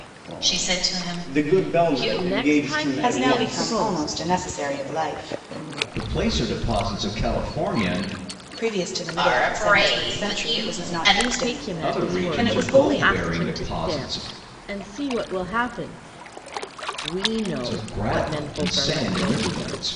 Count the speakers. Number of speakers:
five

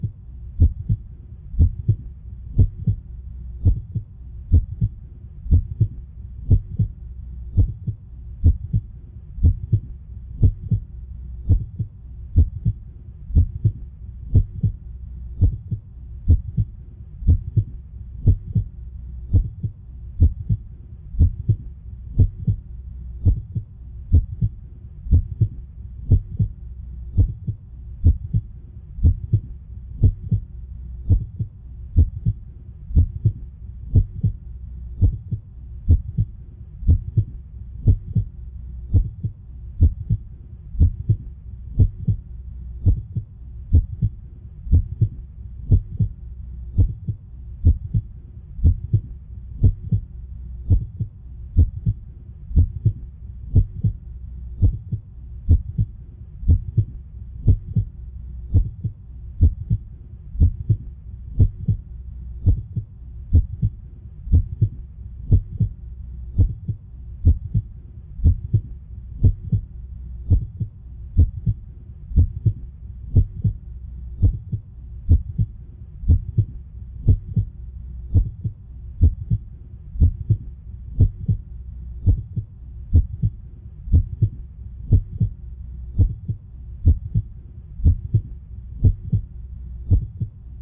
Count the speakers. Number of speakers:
zero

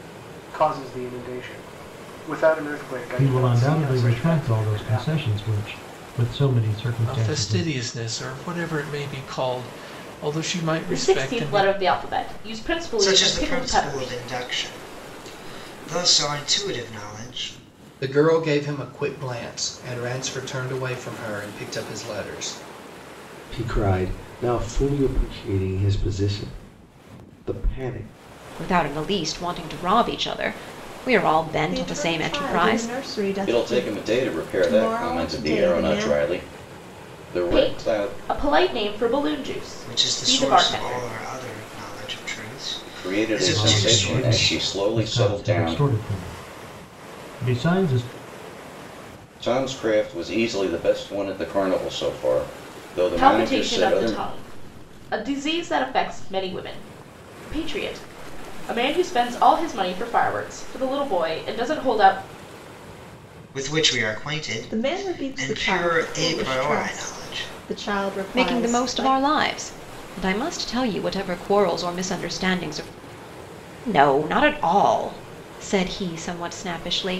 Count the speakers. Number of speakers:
ten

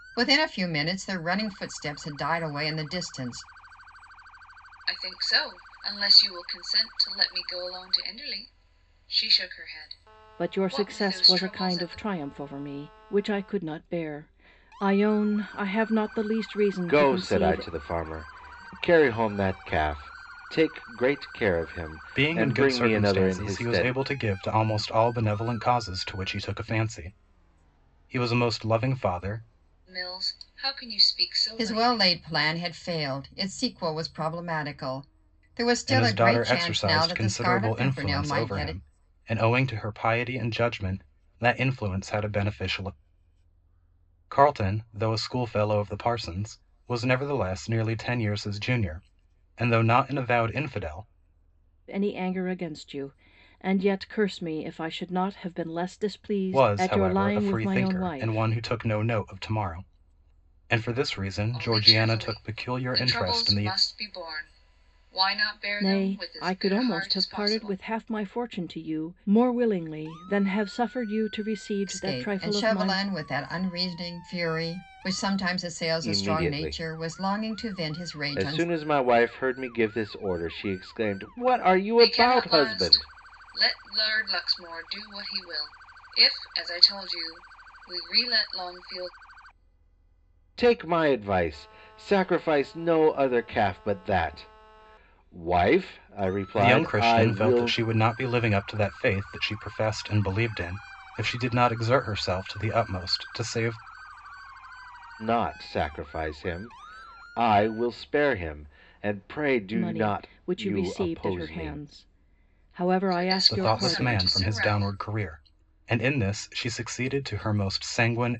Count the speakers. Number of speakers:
five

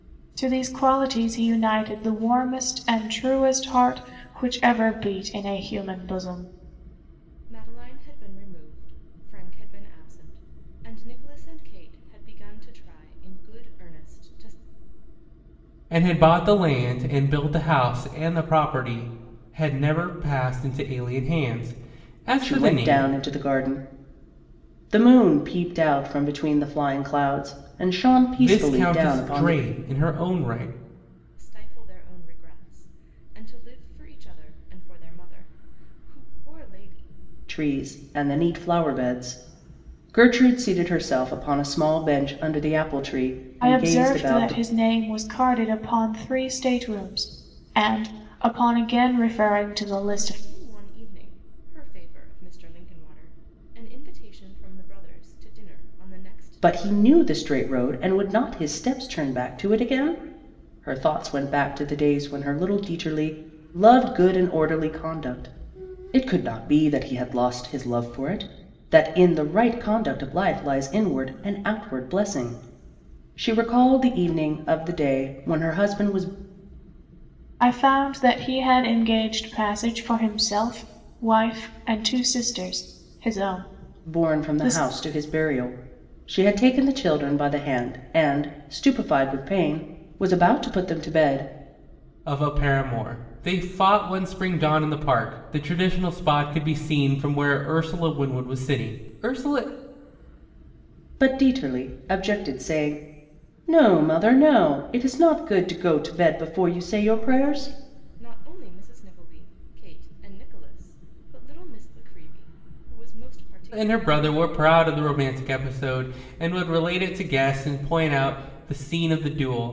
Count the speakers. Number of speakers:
four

